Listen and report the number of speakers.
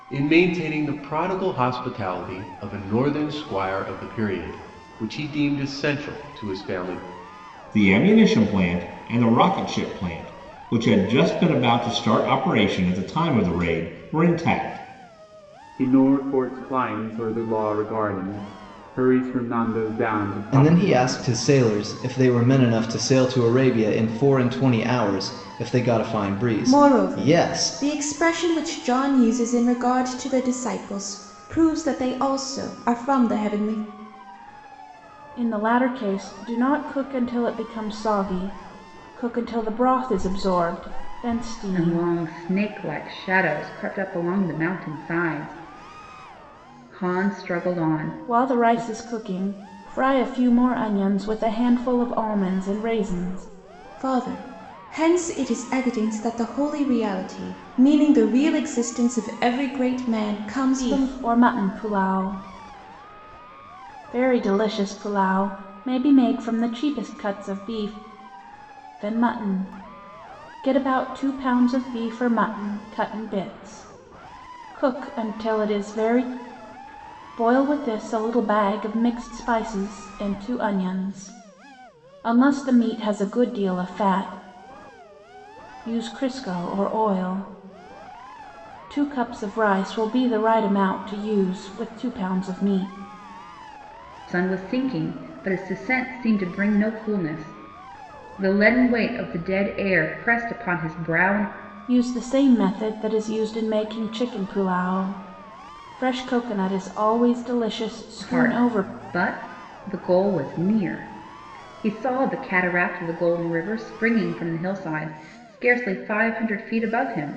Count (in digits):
7